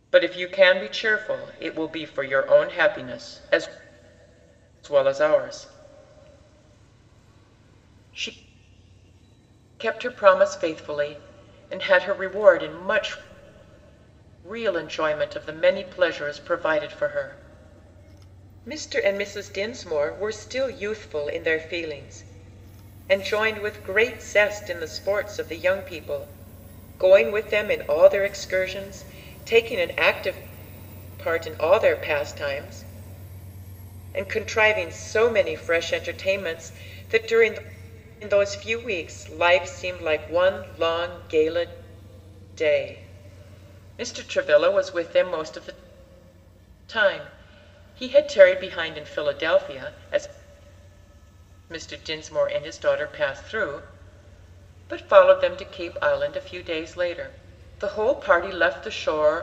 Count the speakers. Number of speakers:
1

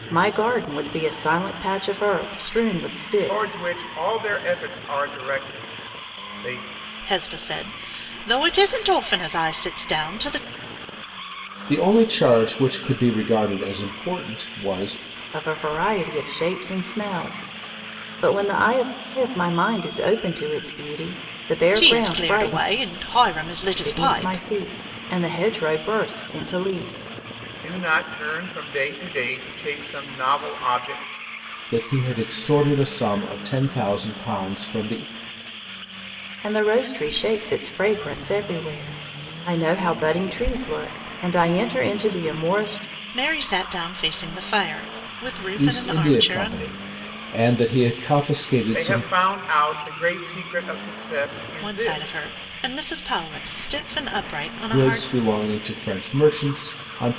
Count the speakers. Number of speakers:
4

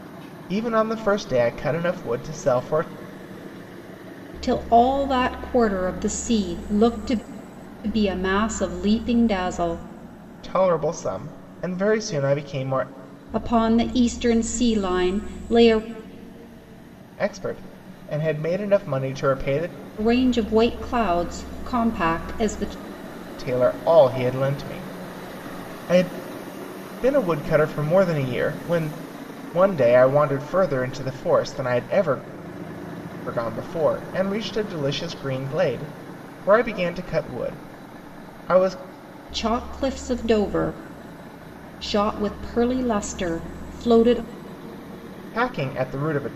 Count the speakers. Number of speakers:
2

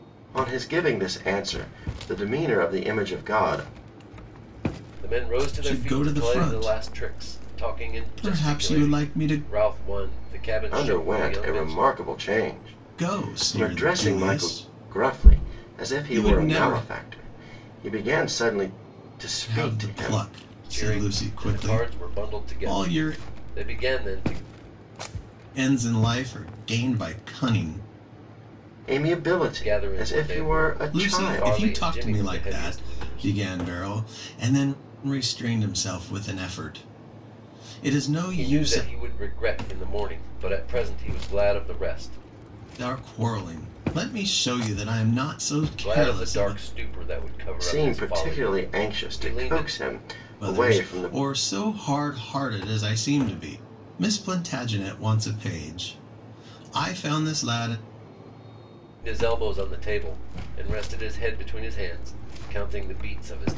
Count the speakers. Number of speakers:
3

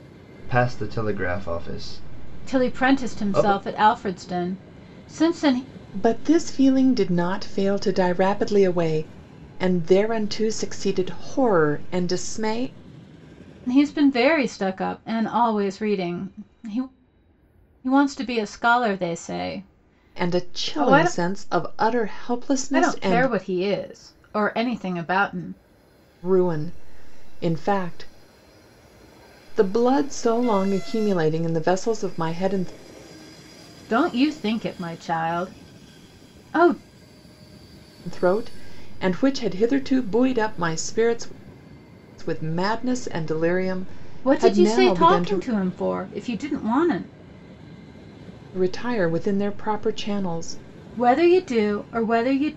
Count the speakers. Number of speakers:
3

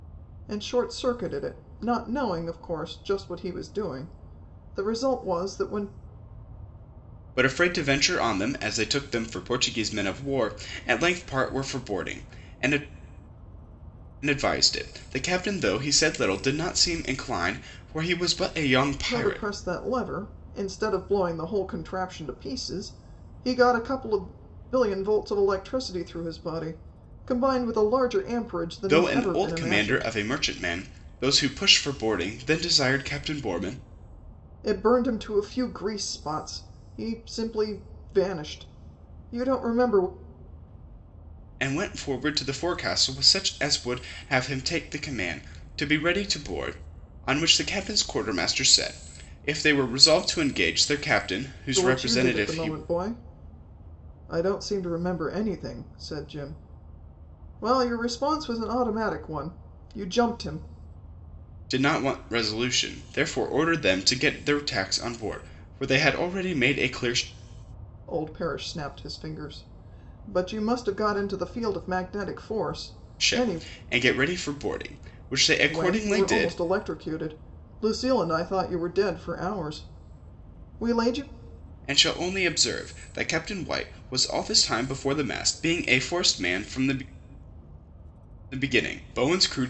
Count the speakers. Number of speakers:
2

